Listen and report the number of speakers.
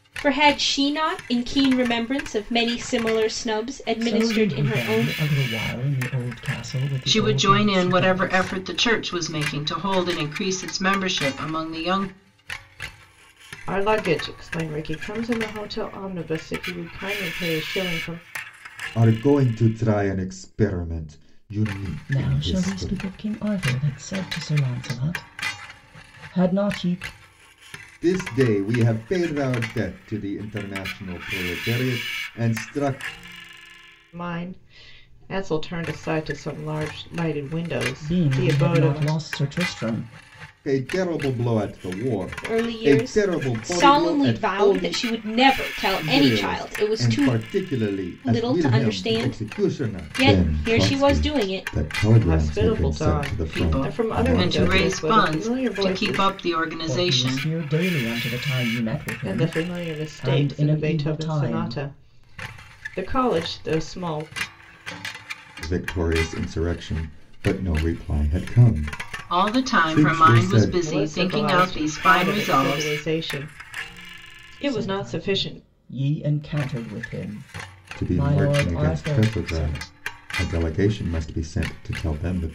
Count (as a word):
five